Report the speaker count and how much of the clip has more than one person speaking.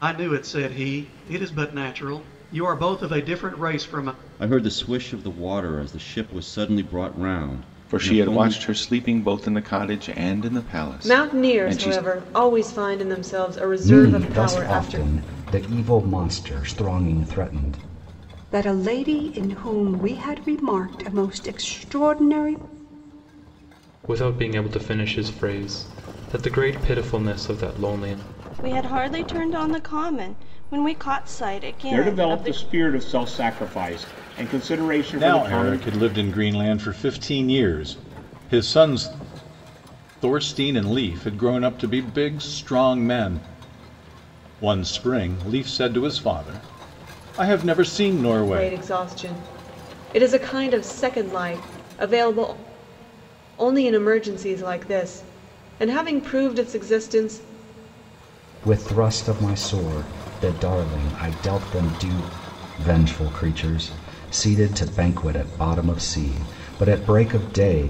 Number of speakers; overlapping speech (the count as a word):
ten, about 7%